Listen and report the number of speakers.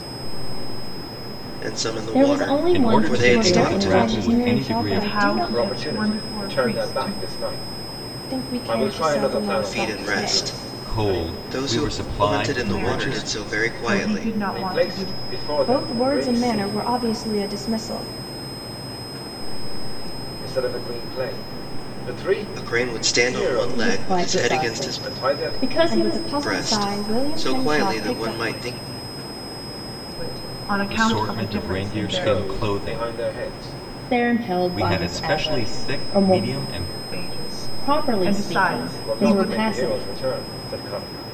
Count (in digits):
7